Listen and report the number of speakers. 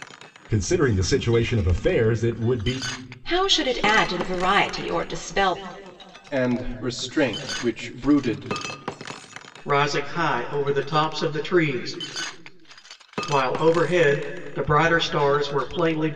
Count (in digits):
4